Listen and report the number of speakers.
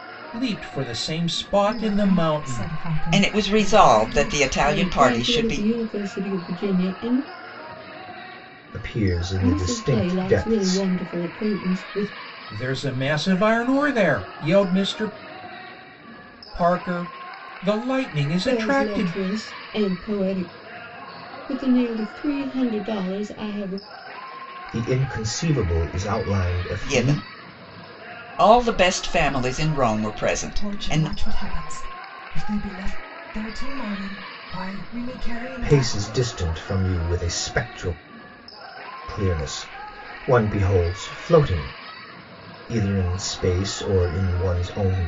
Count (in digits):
5